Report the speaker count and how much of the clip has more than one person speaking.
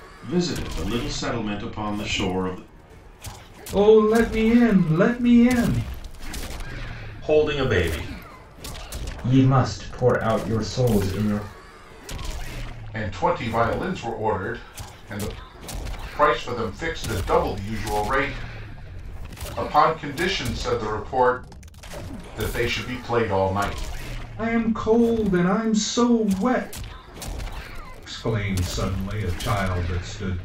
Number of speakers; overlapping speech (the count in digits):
5, no overlap